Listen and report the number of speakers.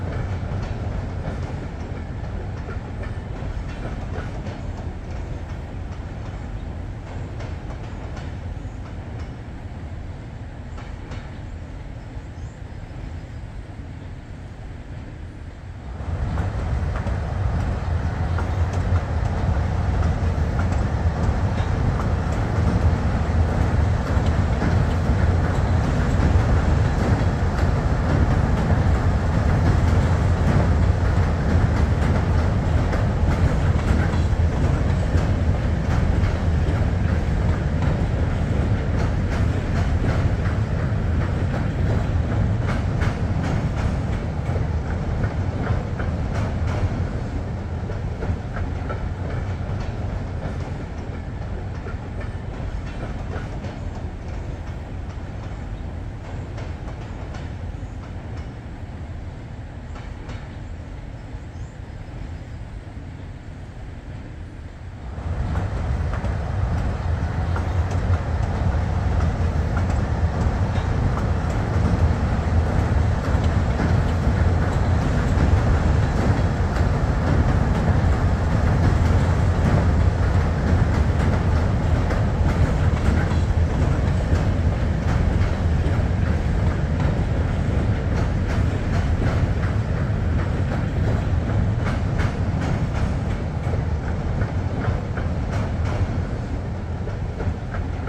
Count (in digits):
0